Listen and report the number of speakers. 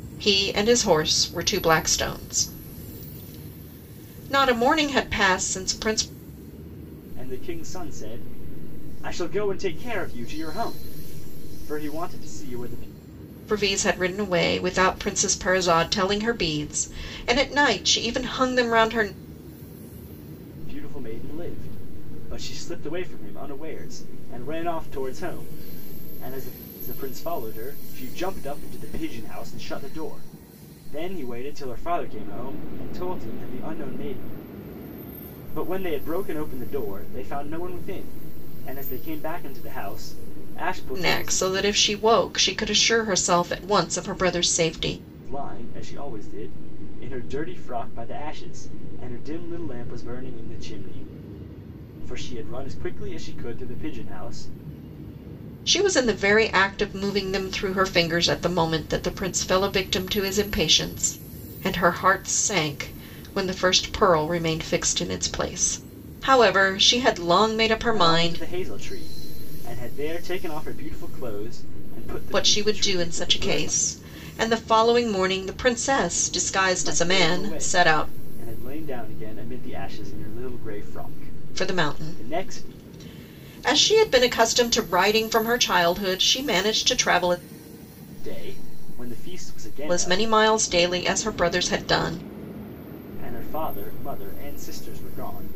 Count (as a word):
two